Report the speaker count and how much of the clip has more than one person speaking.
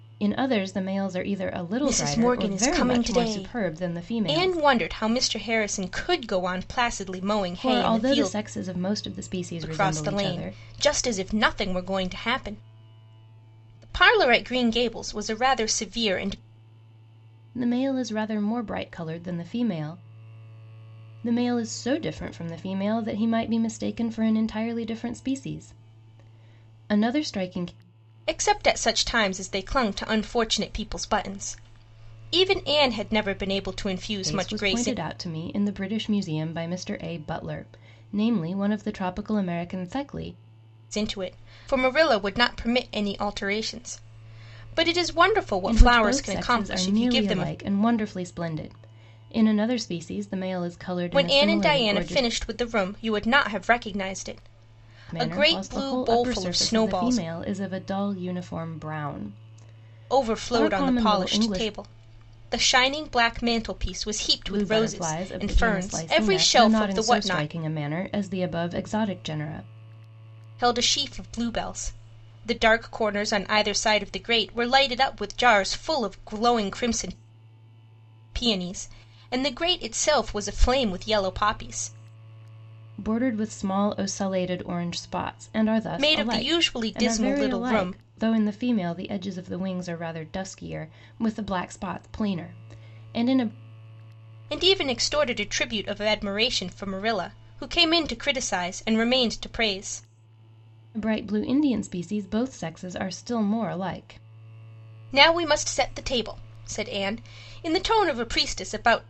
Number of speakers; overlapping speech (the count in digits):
2, about 16%